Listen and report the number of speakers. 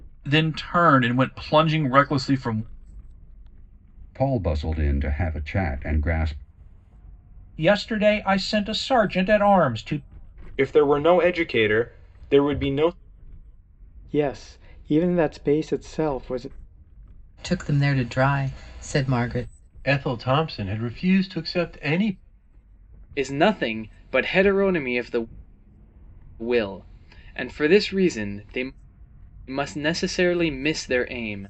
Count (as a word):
eight